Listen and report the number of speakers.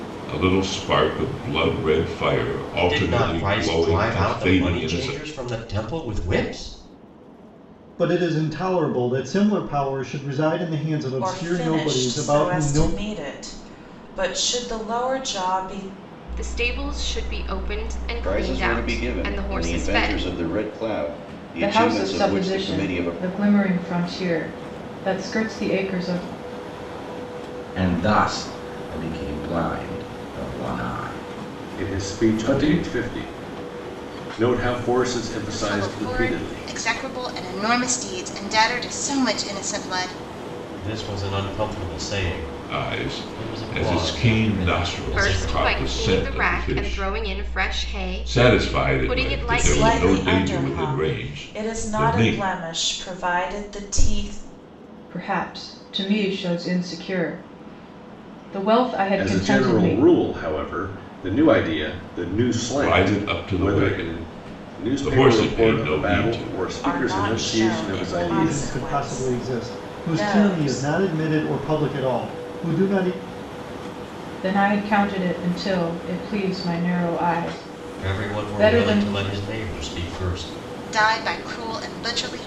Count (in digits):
10